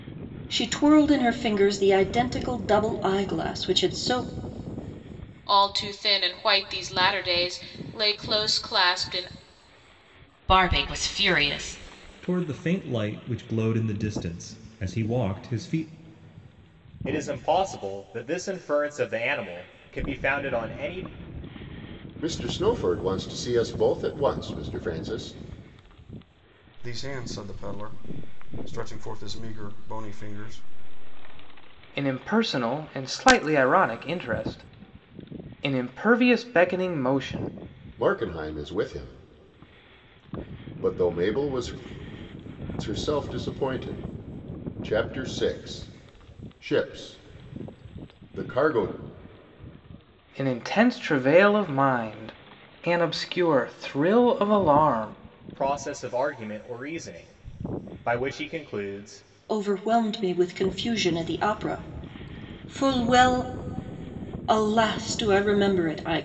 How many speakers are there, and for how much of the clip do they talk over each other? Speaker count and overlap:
8, no overlap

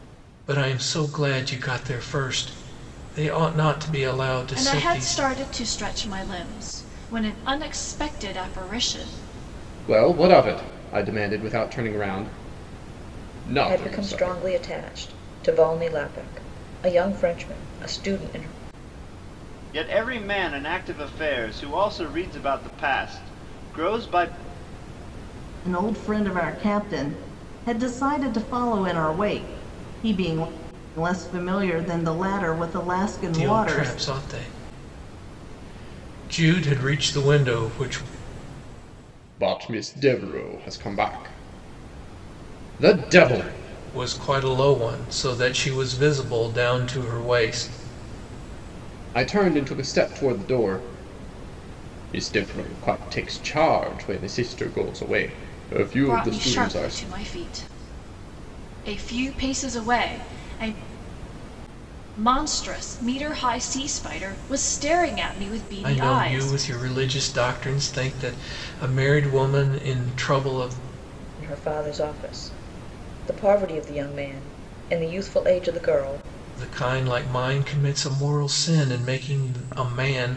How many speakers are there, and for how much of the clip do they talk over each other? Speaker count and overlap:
6, about 5%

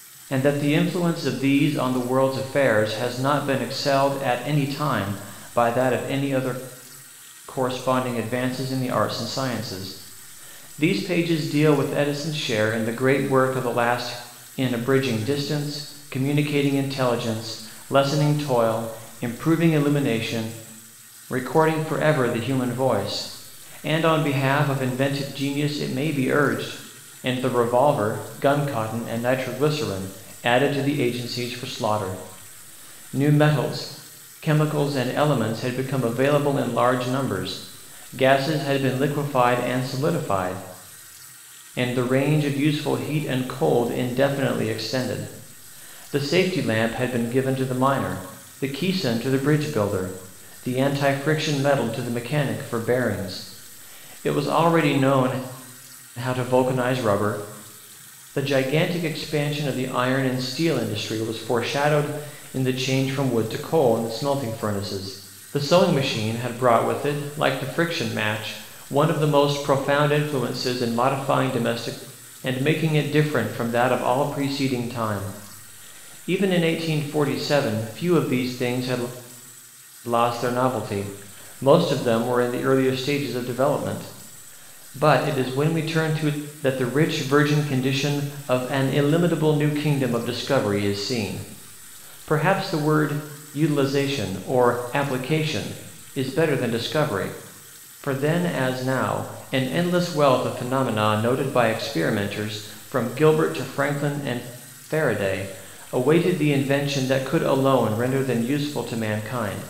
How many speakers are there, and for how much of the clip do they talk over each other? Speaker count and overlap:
1, no overlap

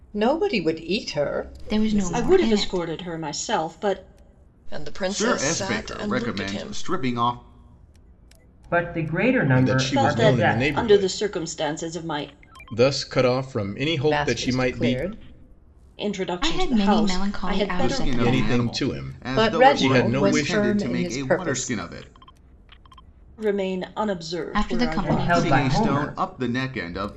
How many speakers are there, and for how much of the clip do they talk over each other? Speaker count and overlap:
7, about 46%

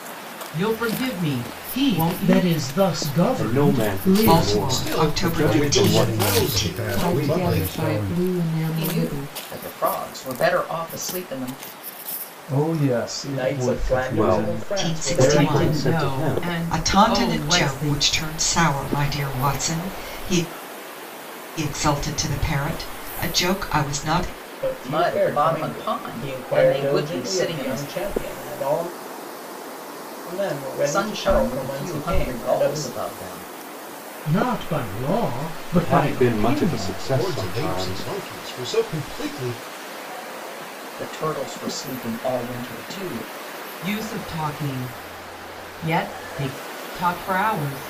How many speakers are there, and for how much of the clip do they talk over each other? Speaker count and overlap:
10, about 39%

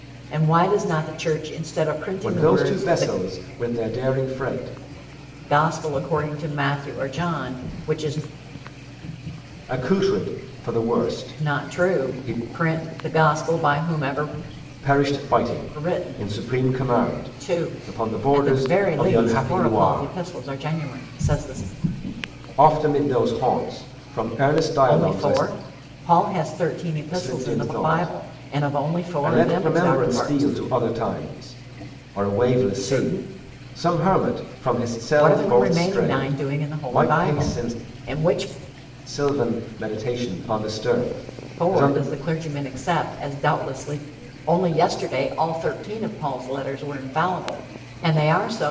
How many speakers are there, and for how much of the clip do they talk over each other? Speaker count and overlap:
2, about 32%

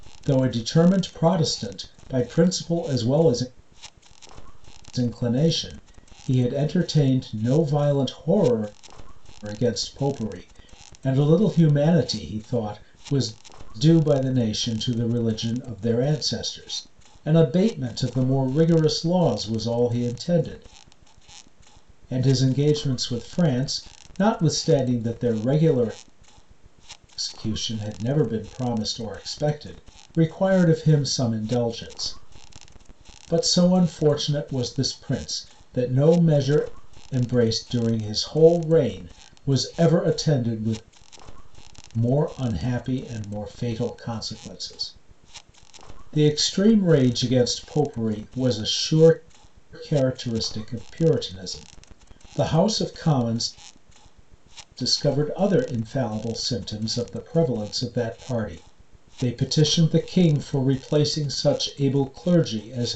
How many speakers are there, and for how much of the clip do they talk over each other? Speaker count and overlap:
1, no overlap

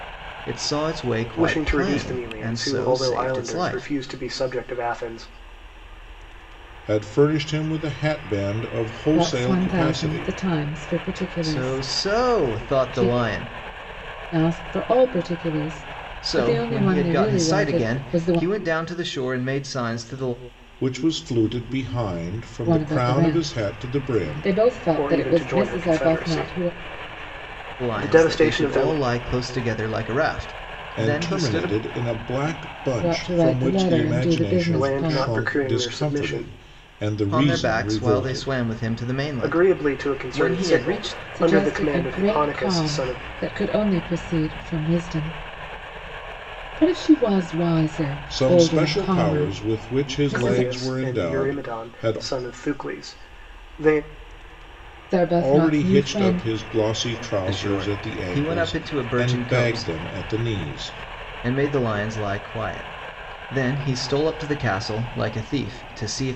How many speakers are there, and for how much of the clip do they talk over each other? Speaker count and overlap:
4, about 45%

